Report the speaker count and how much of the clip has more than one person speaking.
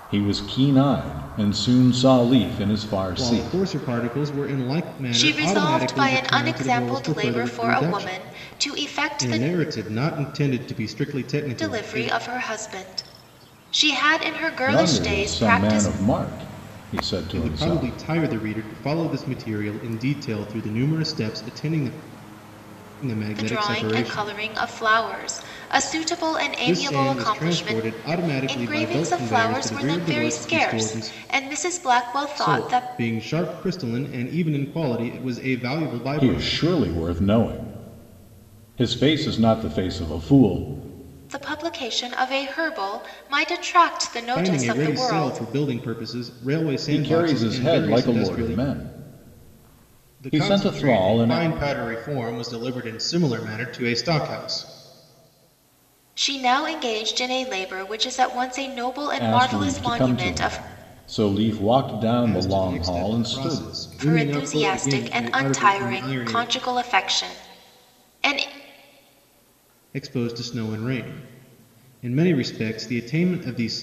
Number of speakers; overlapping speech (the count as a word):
three, about 32%